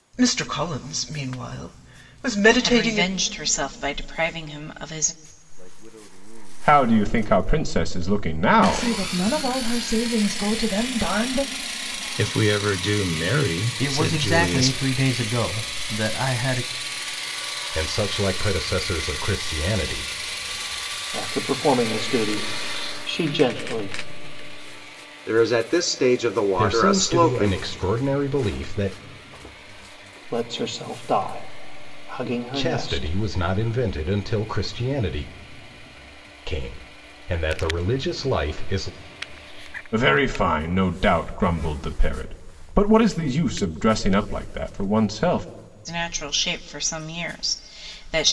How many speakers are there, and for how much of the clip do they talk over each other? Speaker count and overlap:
10, about 10%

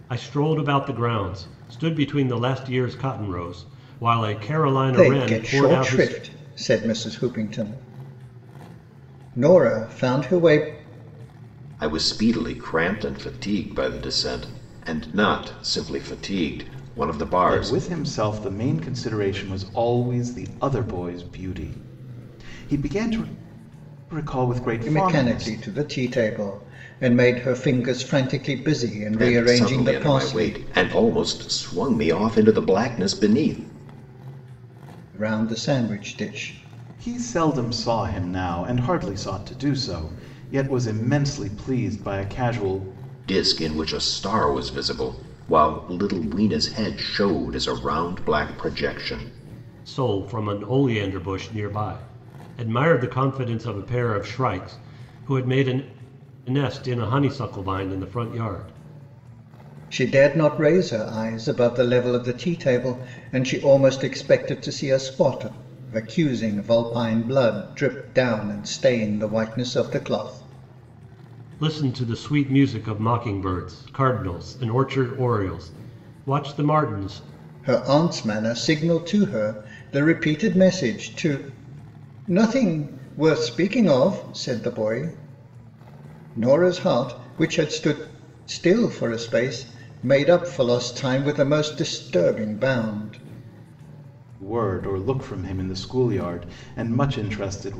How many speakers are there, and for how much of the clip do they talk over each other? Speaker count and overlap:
4, about 4%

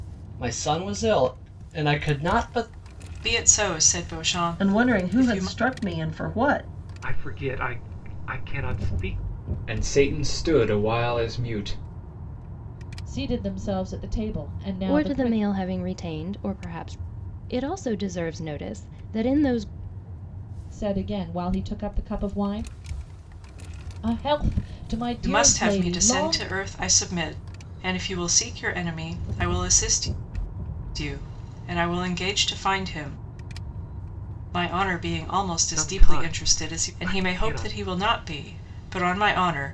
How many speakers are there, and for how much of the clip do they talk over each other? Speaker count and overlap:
7, about 13%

